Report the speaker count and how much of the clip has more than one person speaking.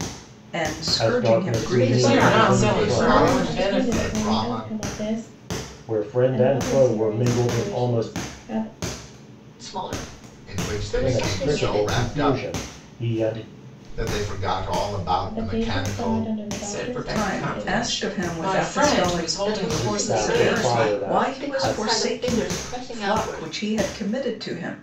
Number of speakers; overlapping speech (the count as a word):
six, about 61%